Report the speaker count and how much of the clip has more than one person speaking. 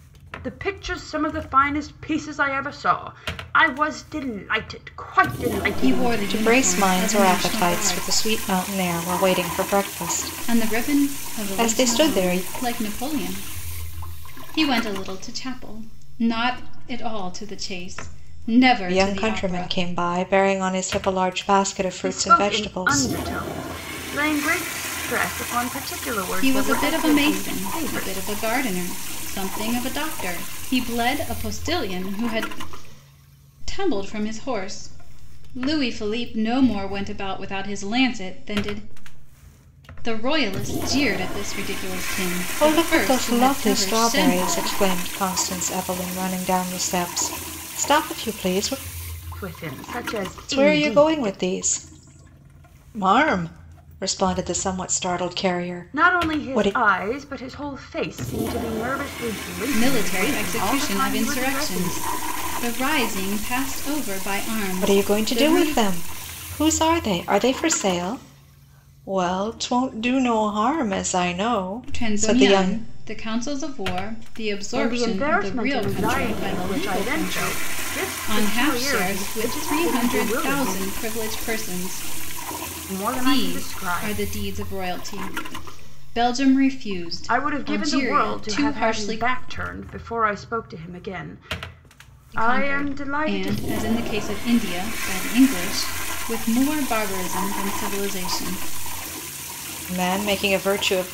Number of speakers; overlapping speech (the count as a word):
three, about 26%